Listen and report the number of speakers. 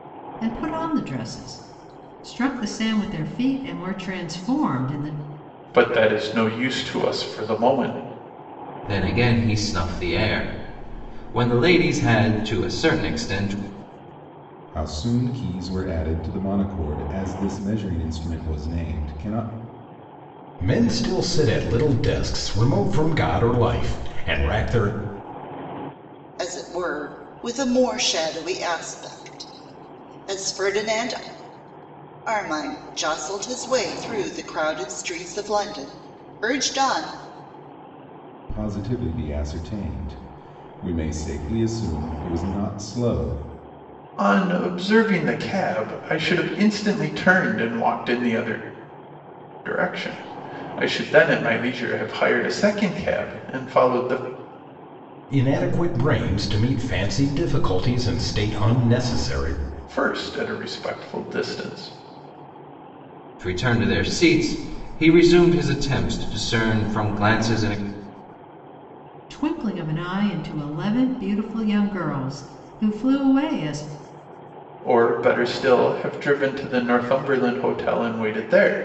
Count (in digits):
6